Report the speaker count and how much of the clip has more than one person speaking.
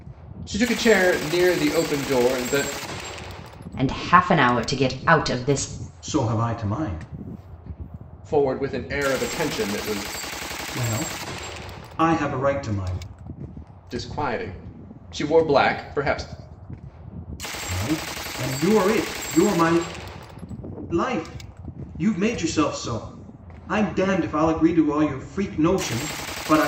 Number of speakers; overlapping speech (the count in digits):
3, no overlap